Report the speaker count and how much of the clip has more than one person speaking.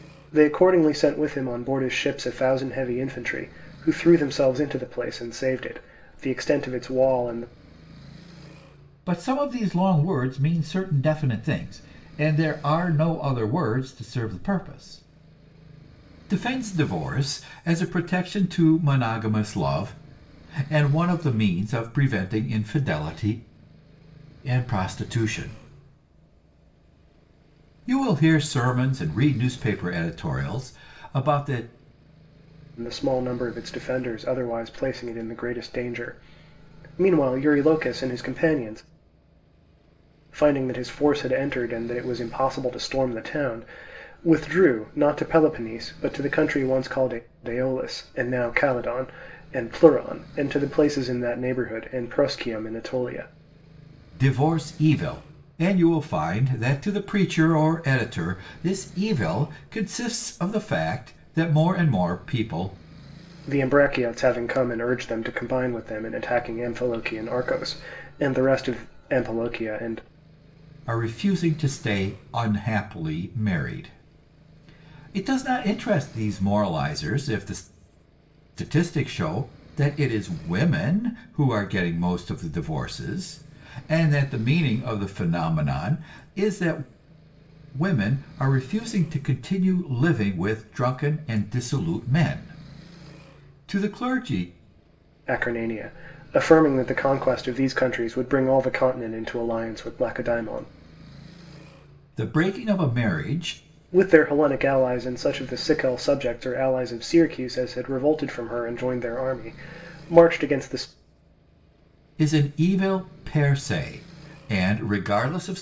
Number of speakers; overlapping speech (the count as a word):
two, no overlap